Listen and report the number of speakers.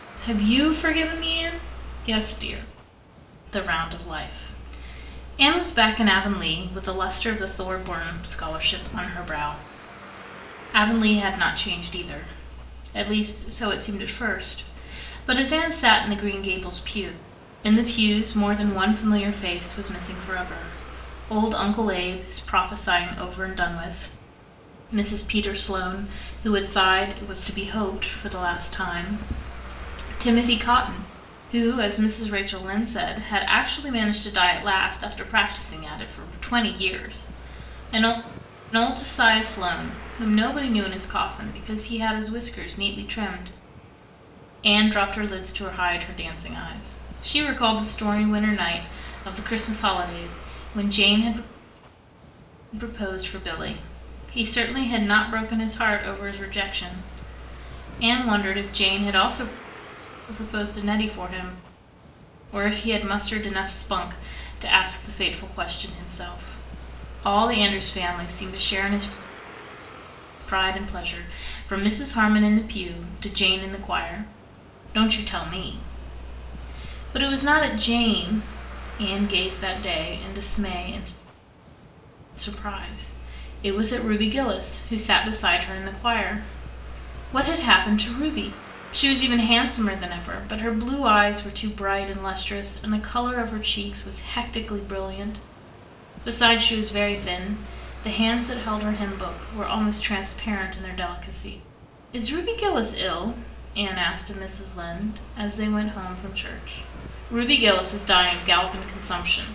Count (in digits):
1